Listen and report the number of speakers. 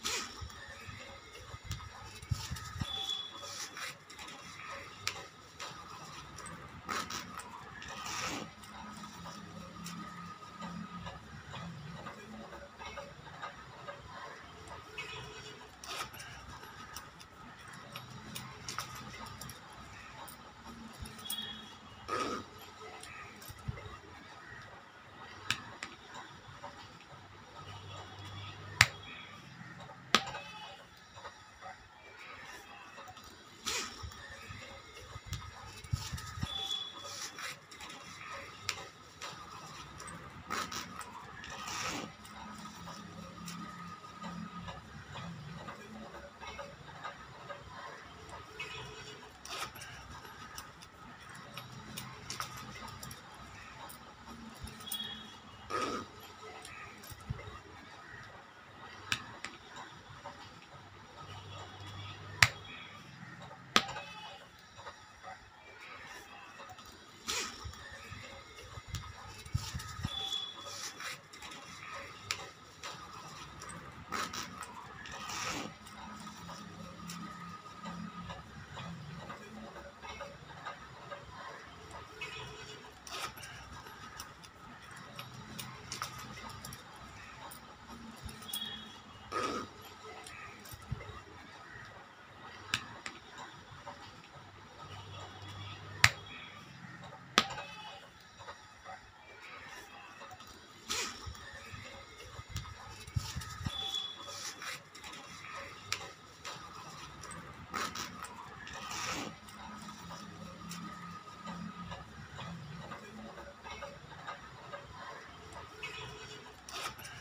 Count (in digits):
0